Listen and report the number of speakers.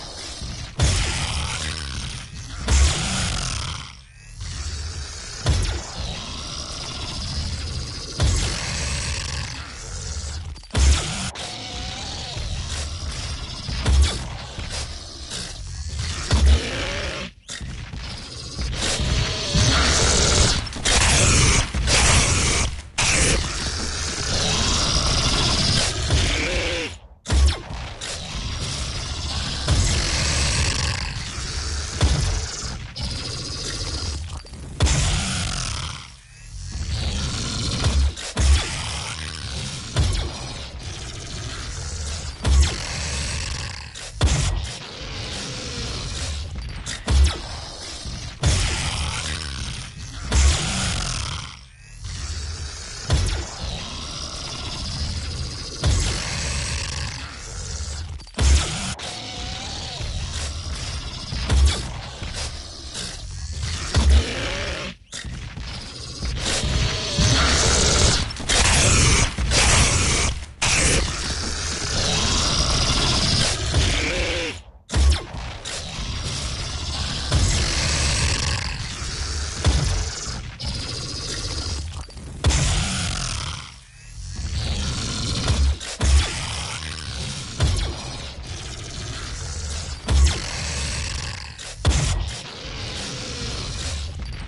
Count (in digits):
0